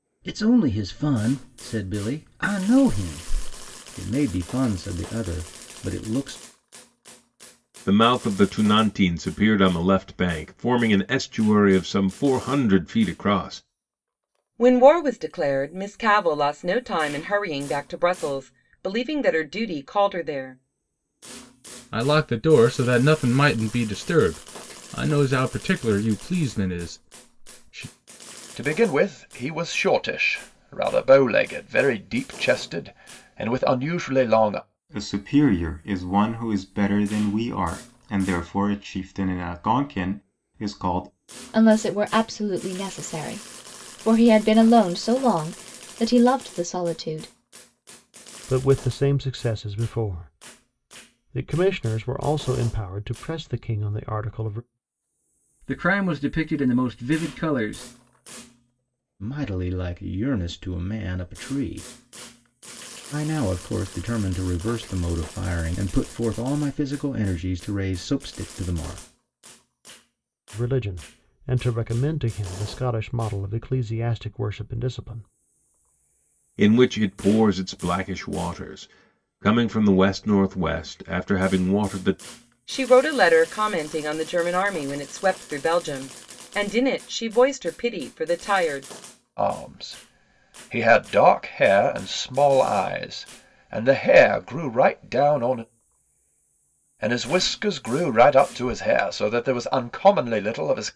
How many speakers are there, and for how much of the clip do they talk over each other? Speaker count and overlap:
nine, no overlap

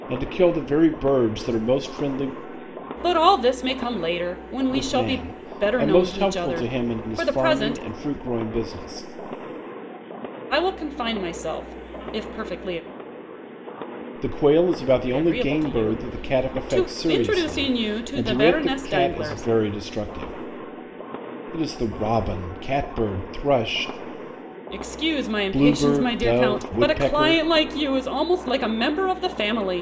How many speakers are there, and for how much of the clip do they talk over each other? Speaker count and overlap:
two, about 30%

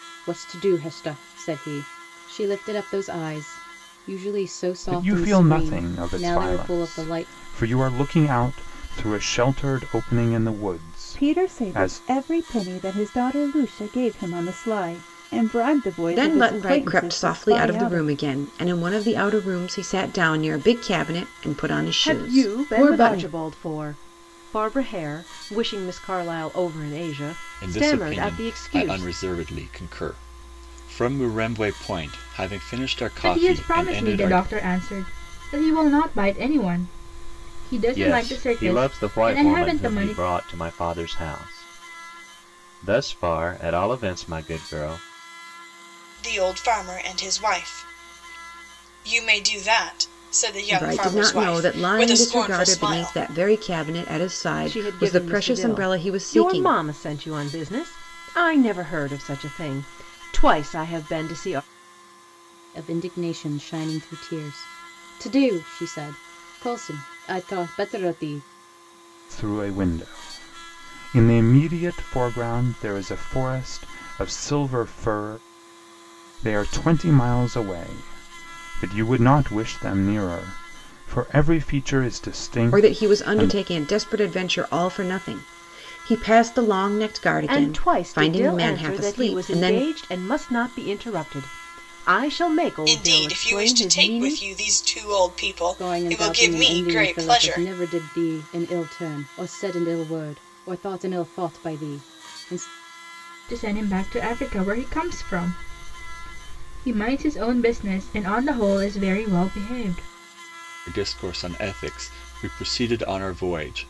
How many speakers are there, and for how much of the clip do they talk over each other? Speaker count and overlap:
nine, about 21%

